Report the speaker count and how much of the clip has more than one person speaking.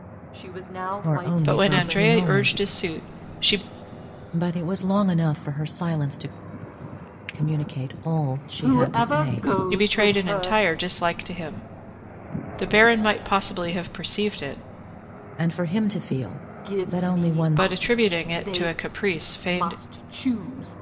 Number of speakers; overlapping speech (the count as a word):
three, about 29%